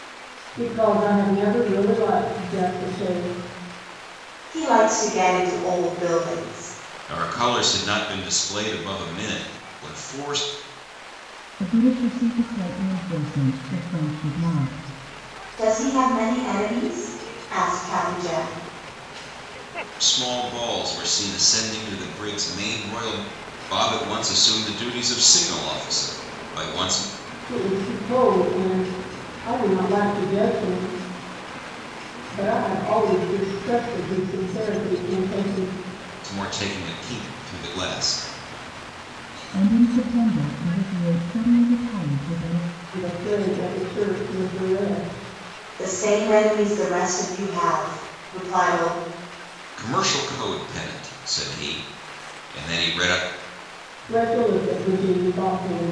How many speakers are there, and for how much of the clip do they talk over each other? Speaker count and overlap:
four, no overlap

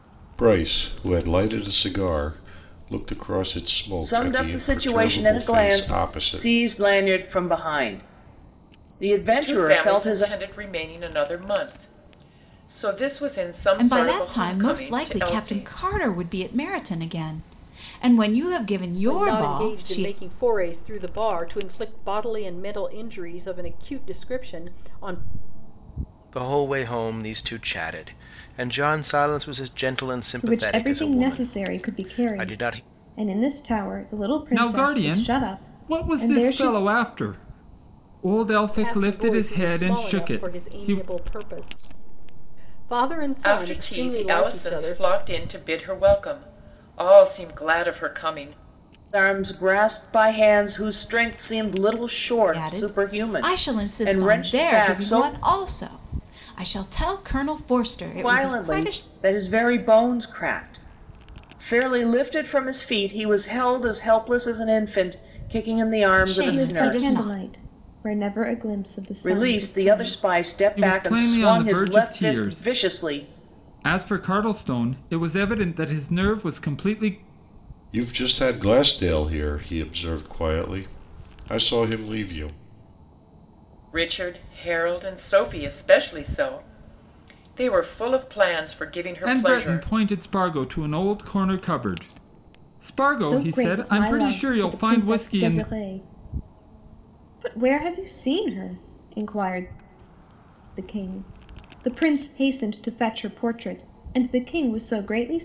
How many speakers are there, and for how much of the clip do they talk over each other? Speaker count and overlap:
eight, about 26%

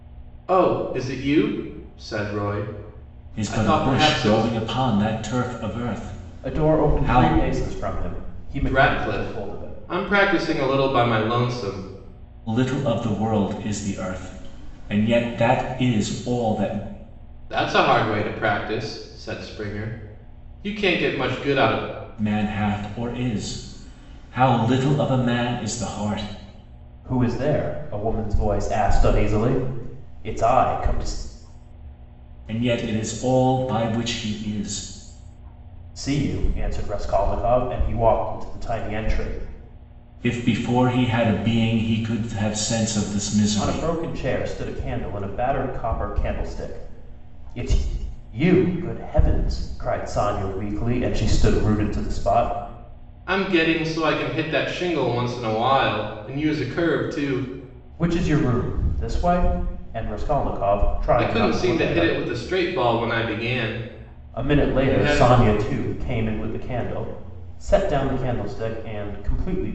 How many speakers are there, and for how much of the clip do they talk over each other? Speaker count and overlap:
three, about 8%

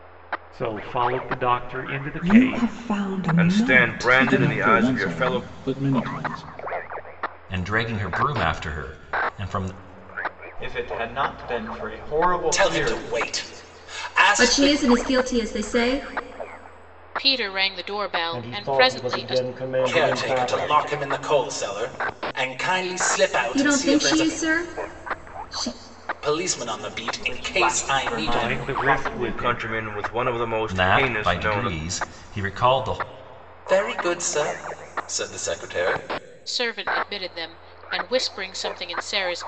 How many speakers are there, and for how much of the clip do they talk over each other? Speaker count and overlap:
ten, about 26%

